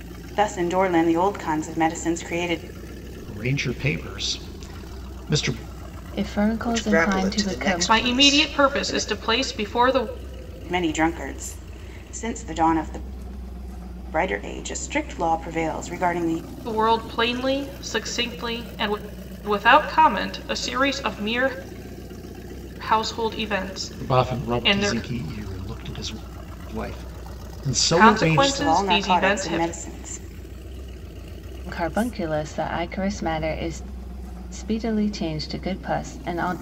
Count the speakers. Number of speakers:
five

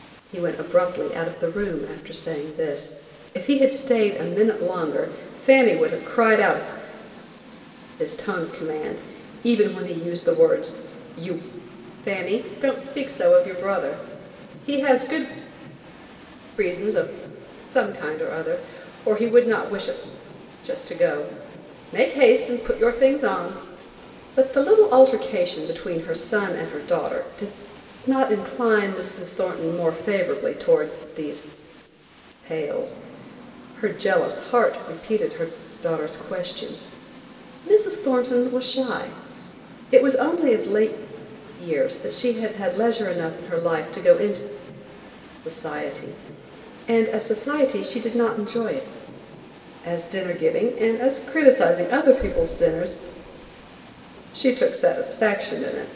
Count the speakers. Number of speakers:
one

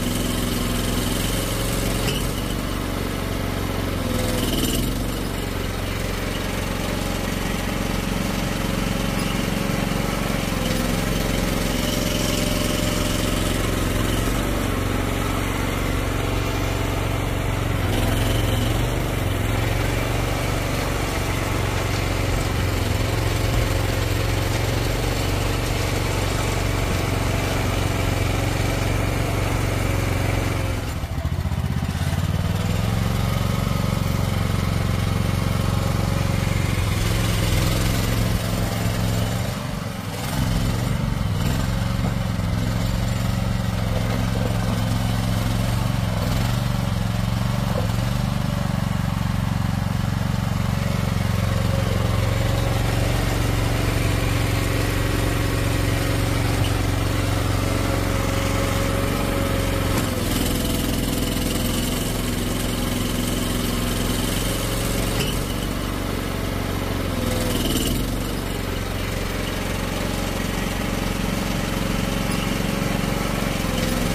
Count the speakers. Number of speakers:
zero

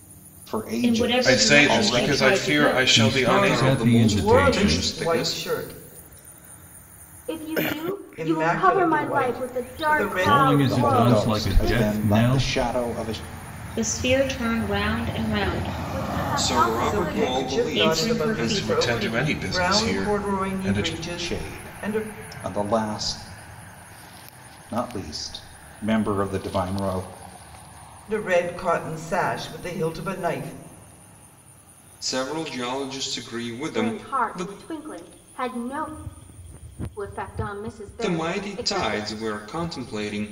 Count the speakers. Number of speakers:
seven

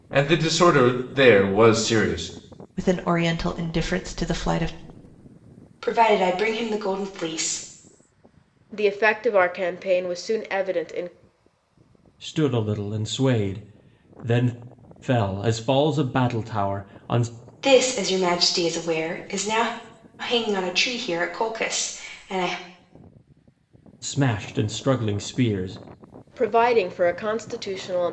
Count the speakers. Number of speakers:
five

